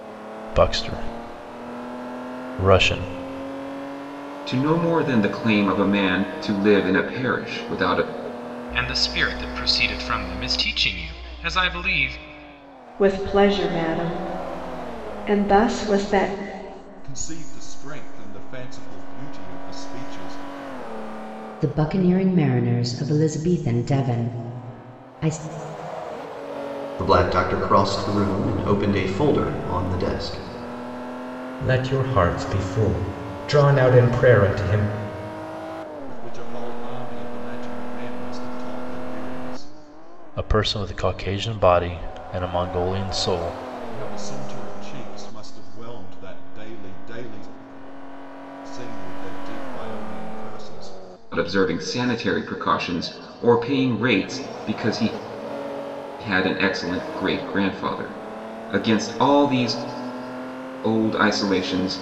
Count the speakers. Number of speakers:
eight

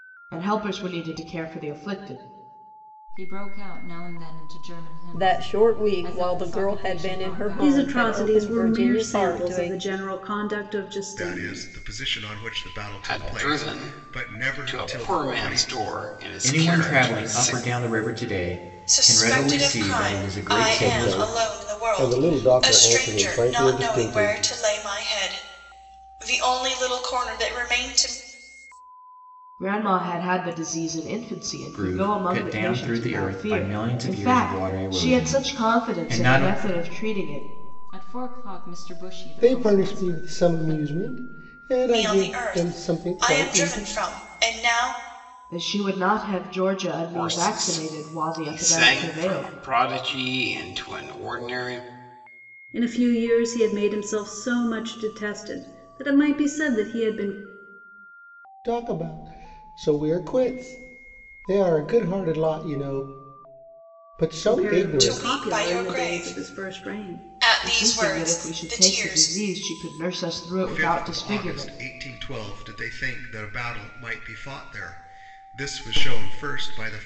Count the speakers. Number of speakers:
nine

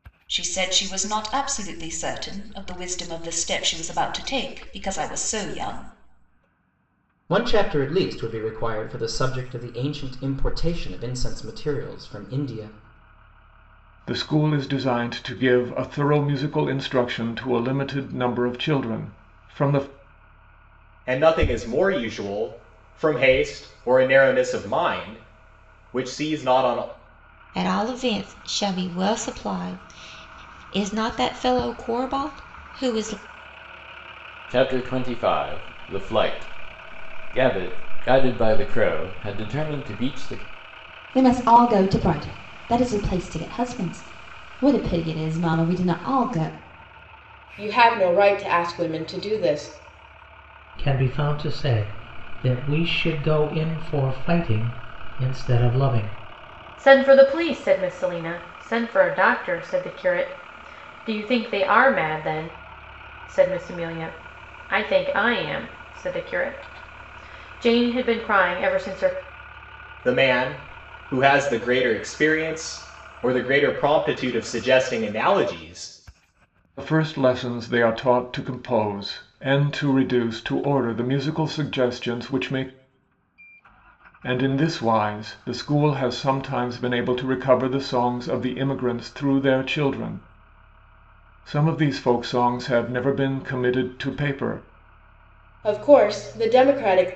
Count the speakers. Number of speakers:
ten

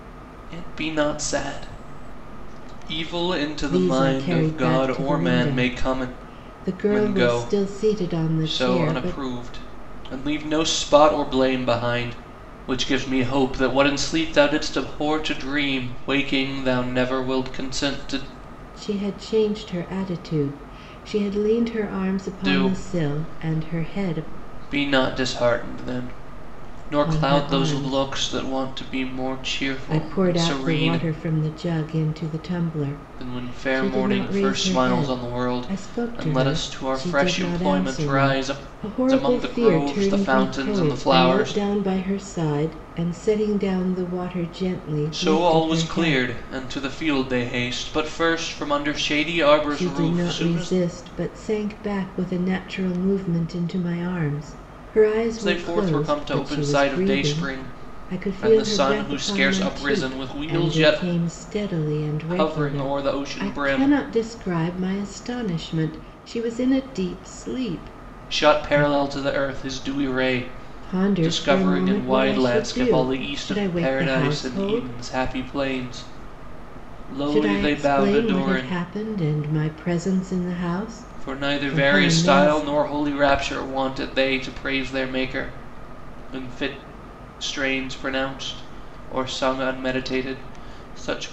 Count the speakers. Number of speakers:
two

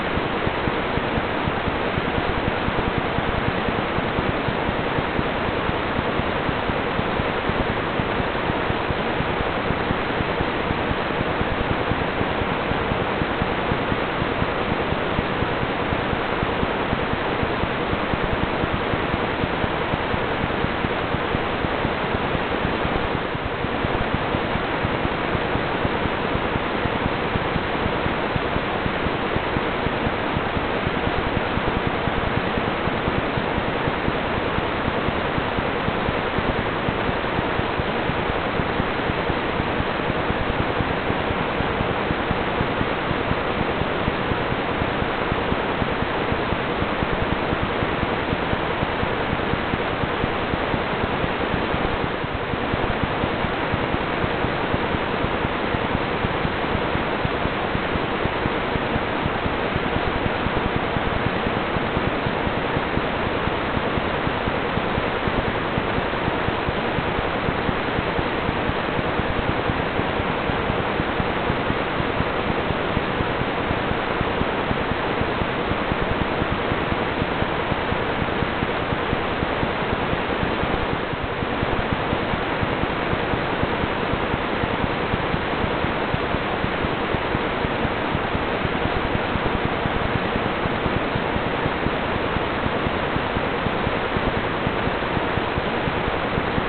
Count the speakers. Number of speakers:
zero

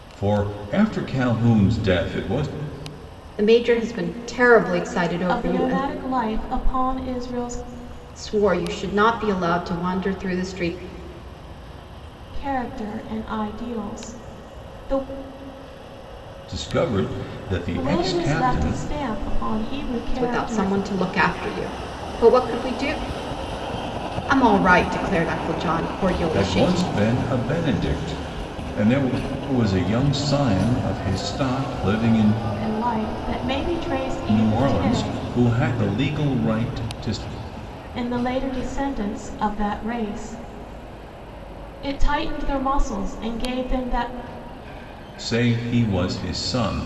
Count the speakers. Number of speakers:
three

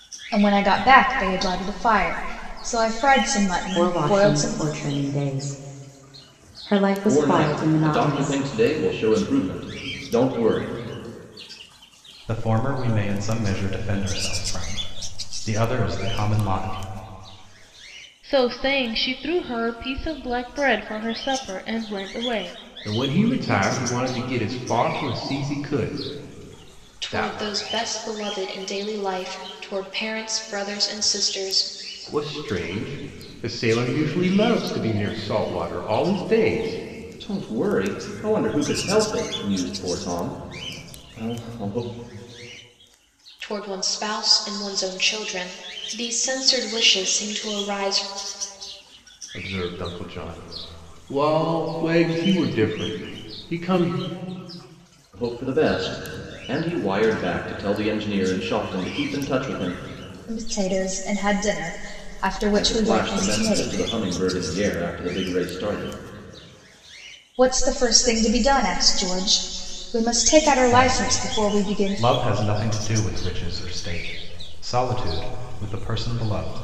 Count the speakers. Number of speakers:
seven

